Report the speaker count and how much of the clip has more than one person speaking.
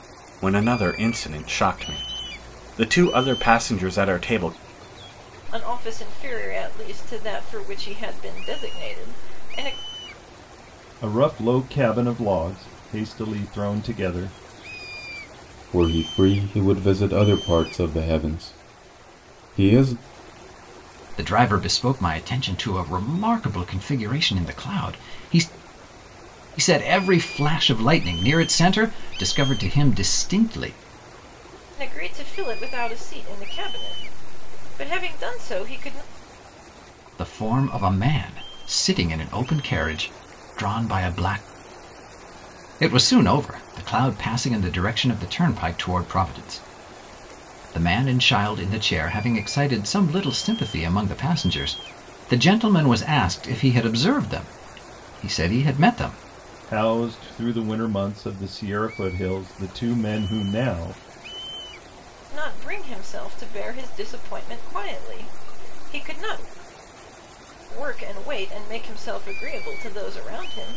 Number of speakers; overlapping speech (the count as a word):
five, no overlap